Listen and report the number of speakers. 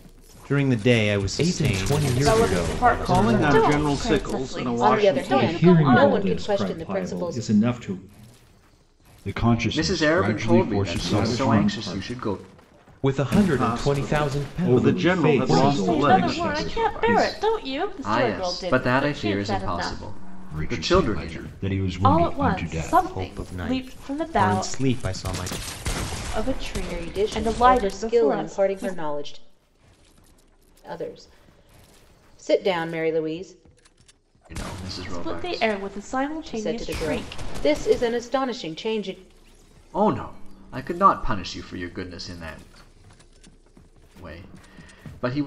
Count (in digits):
9